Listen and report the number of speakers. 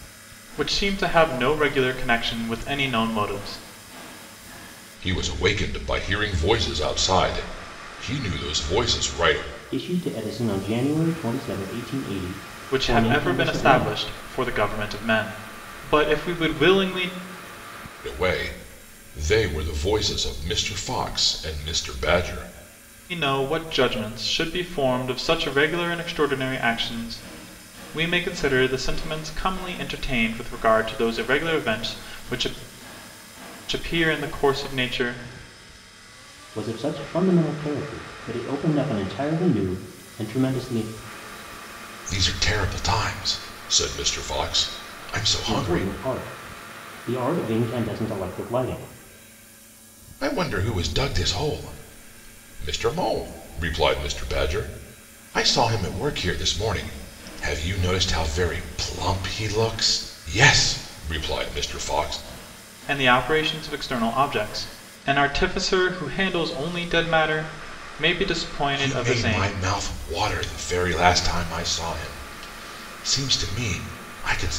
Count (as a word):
three